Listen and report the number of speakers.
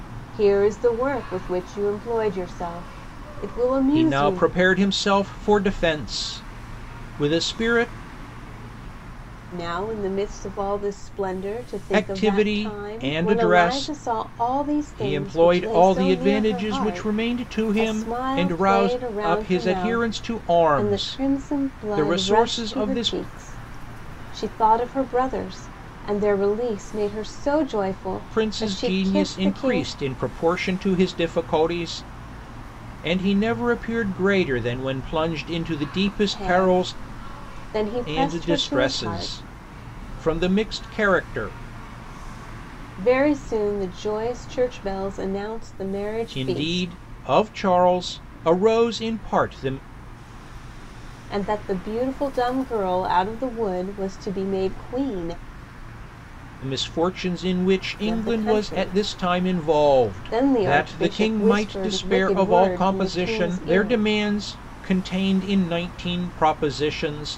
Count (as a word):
two